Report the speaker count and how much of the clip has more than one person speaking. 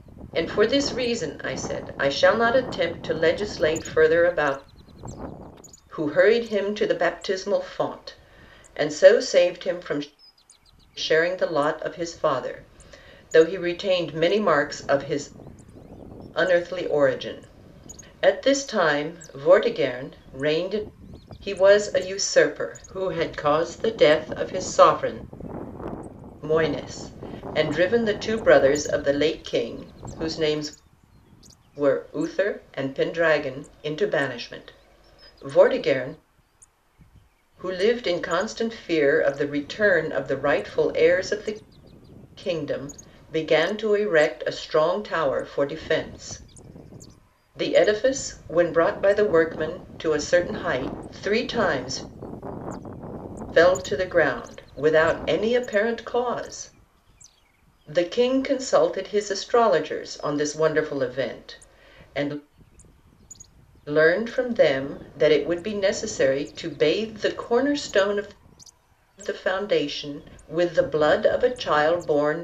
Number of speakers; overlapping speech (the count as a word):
one, no overlap